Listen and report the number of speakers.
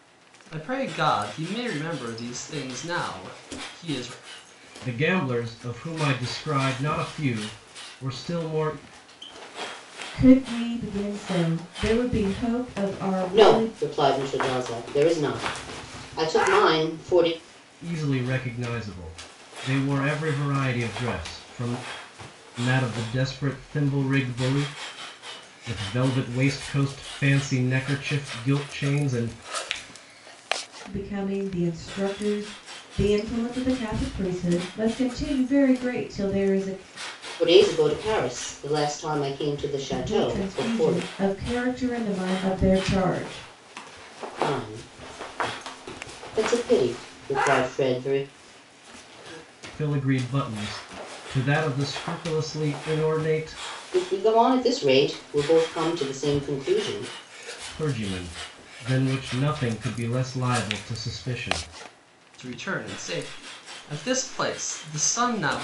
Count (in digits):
4